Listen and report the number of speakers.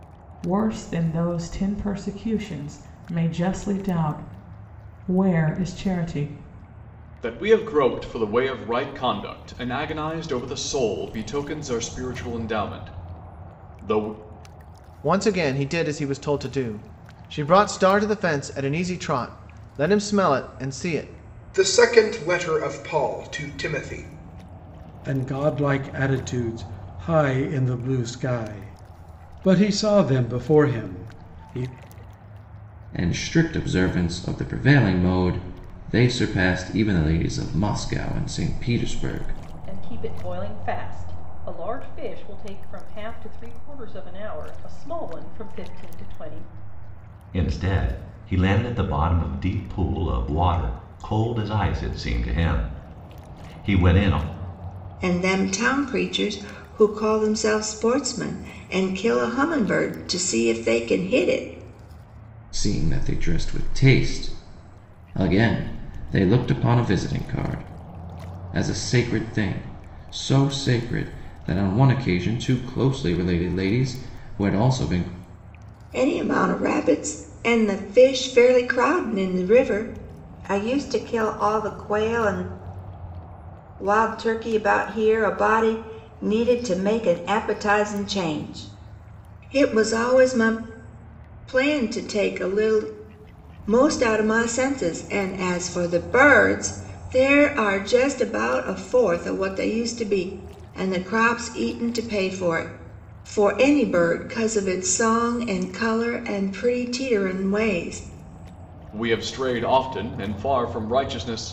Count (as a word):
nine